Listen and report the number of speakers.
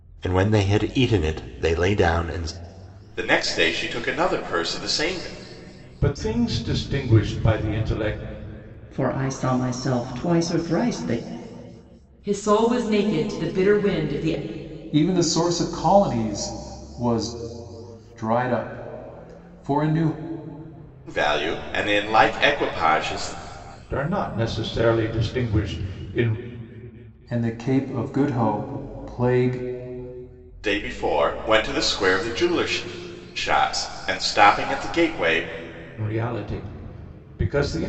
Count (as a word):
six